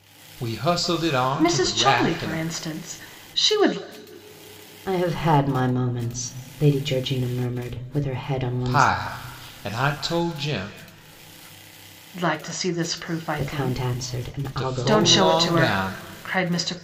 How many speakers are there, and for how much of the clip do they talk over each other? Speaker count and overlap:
three, about 21%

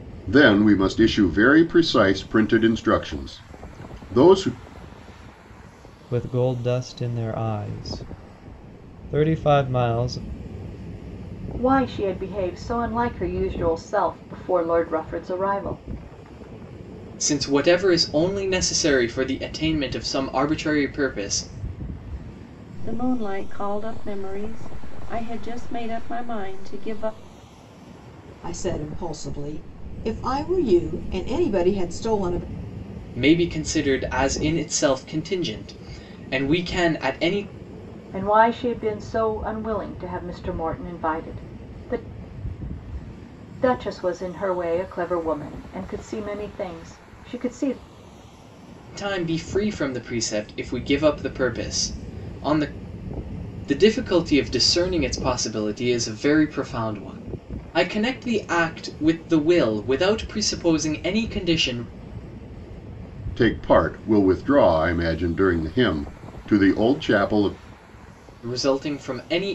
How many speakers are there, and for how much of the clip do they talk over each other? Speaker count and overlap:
six, no overlap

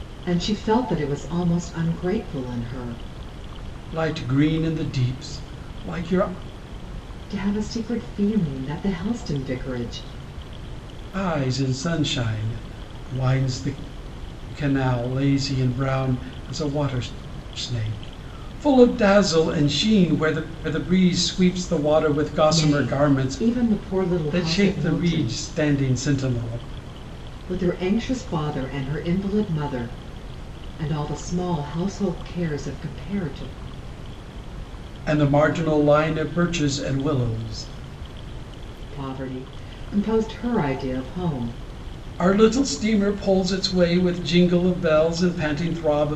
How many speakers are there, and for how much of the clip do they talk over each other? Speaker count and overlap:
two, about 4%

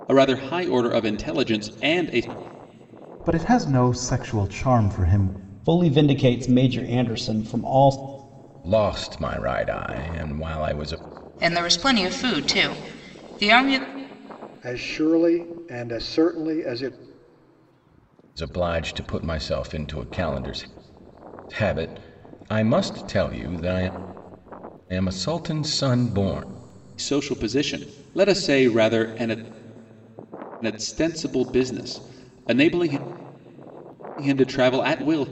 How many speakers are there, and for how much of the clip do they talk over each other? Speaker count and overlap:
six, no overlap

